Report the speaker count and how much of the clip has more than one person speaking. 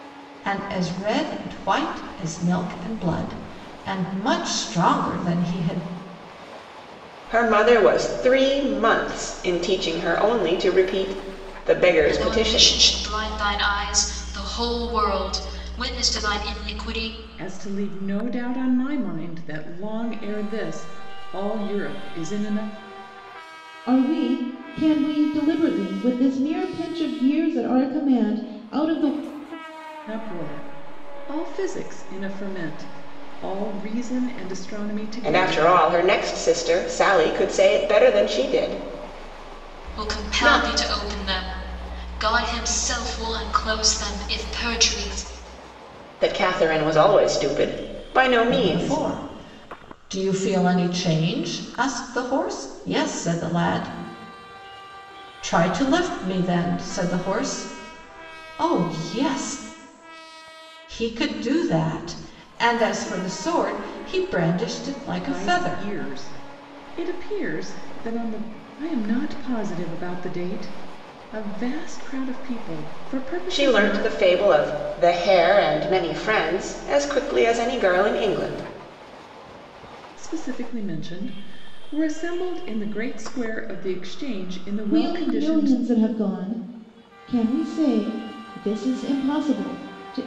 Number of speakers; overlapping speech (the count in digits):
5, about 5%